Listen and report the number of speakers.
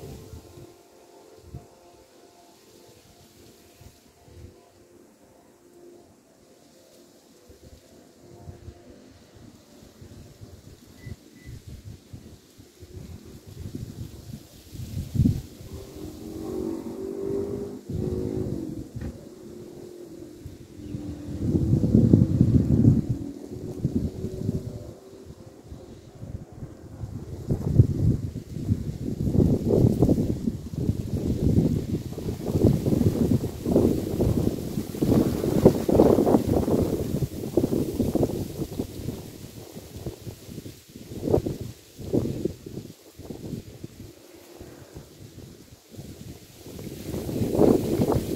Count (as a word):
zero